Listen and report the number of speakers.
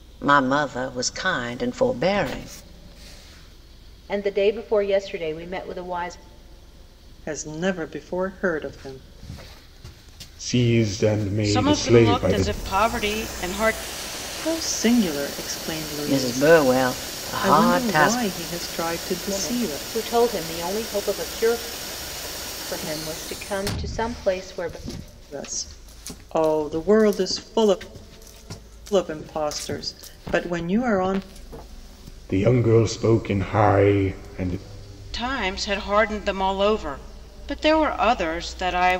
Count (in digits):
5